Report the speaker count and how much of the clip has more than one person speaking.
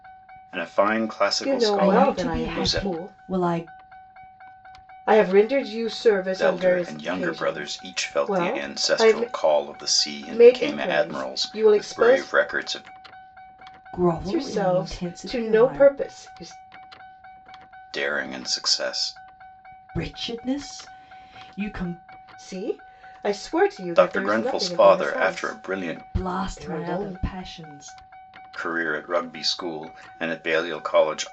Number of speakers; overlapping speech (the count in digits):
3, about 37%